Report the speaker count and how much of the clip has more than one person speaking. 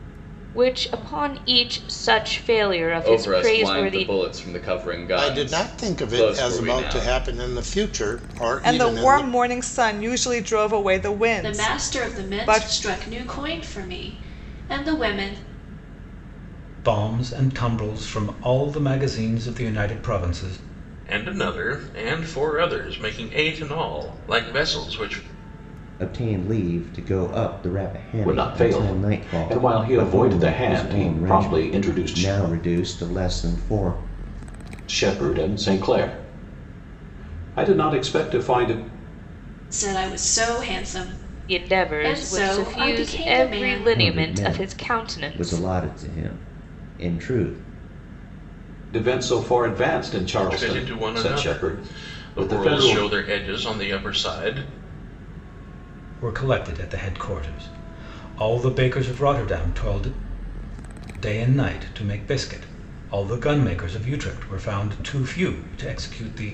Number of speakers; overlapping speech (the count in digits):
9, about 24%